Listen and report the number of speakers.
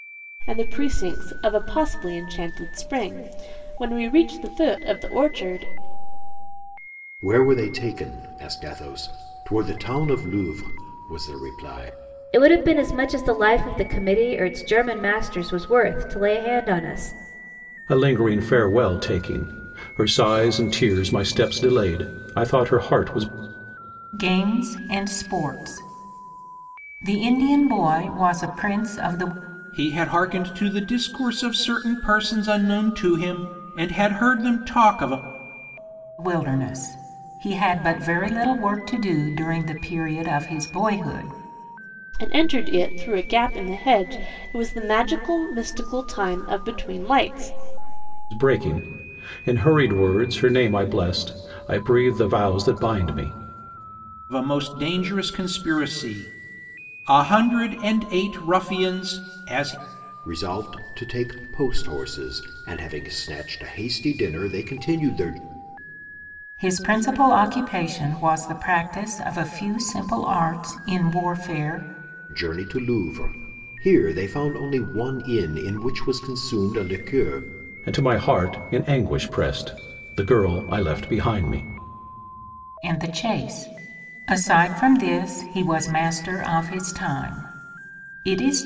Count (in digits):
6